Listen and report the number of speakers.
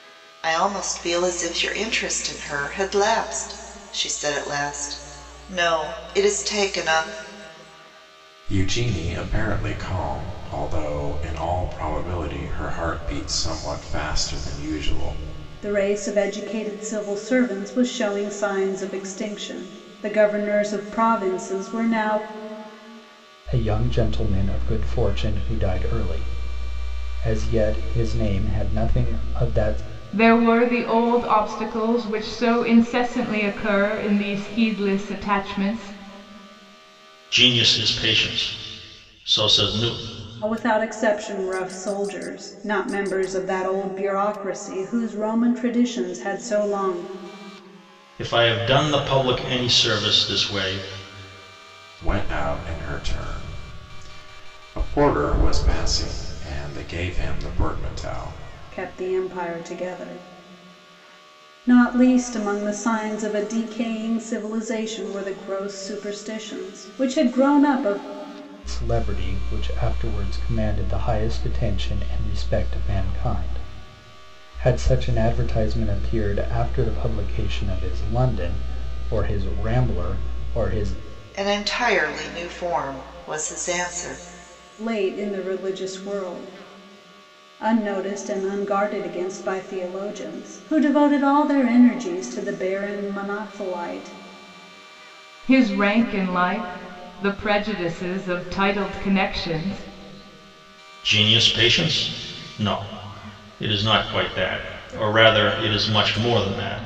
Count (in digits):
6